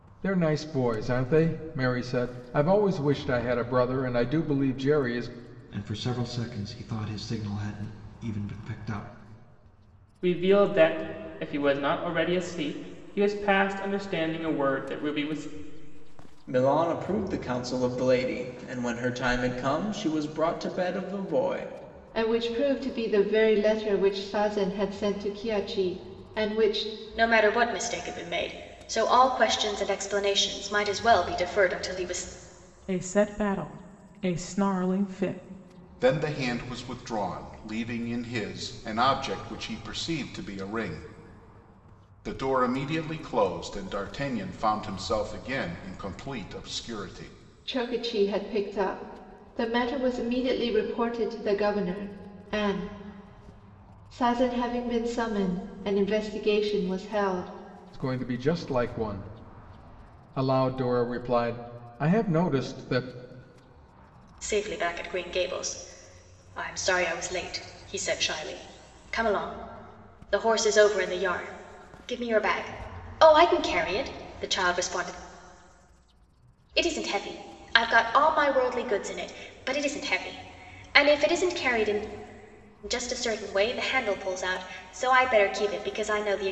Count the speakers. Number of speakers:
8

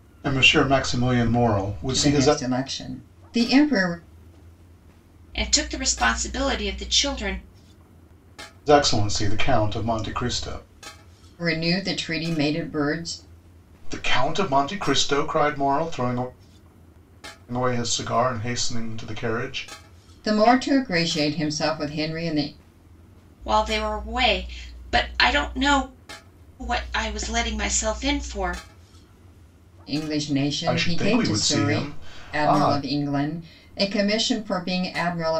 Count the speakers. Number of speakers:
3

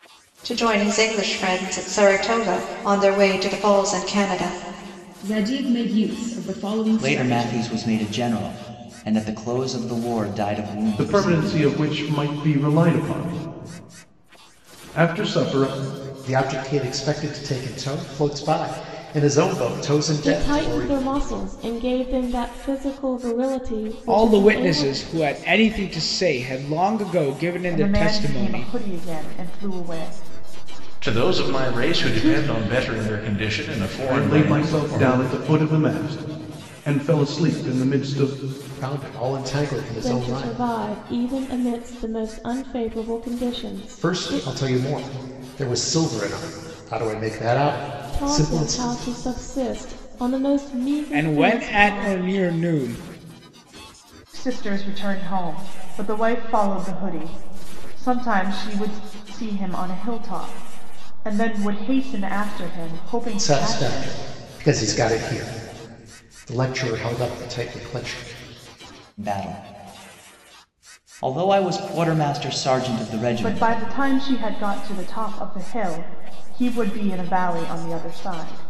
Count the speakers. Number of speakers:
9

